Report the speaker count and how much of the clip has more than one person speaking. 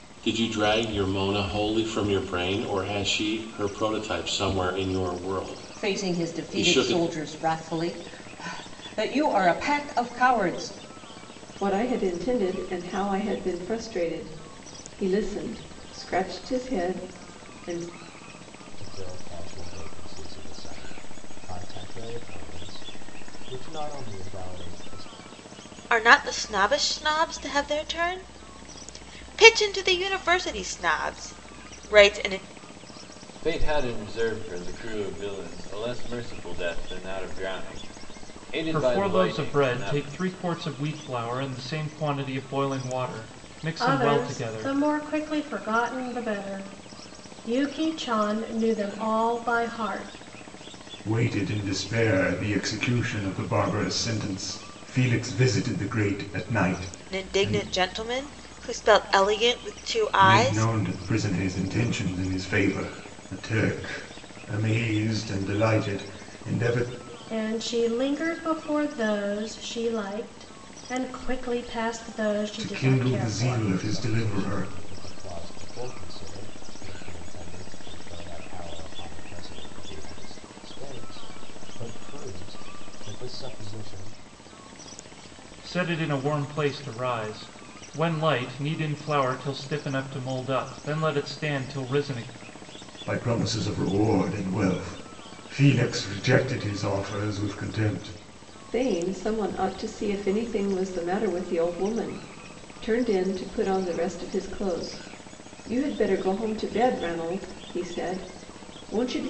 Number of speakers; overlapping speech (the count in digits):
9, about 6%